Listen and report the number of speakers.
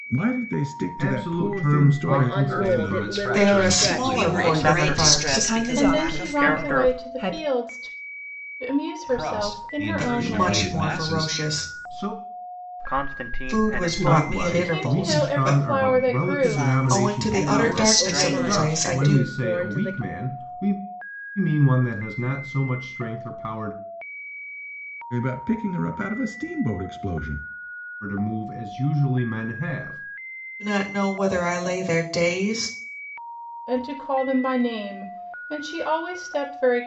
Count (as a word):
nine